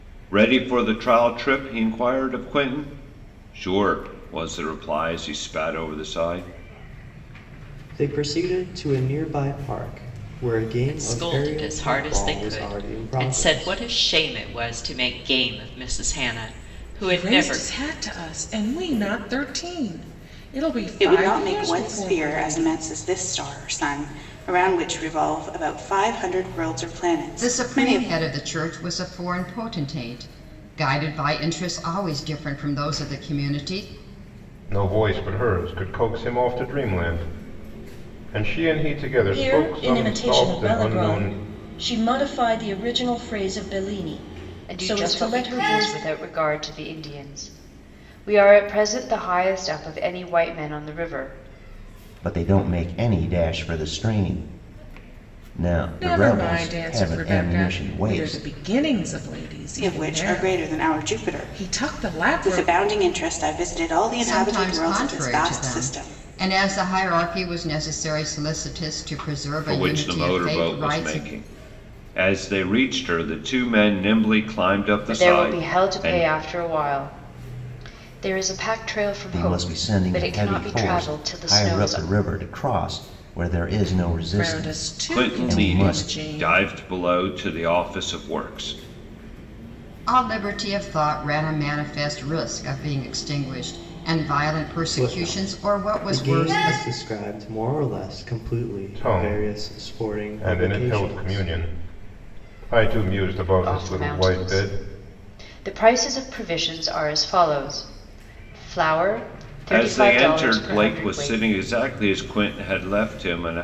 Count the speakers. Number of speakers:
10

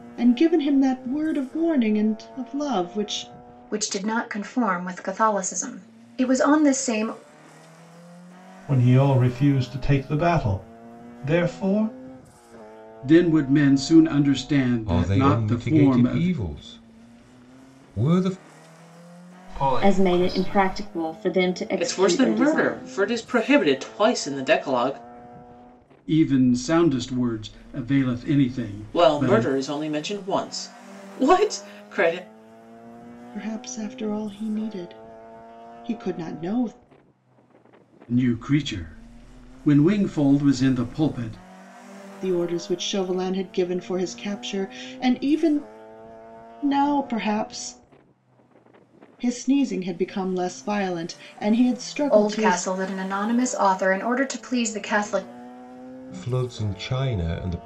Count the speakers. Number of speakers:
8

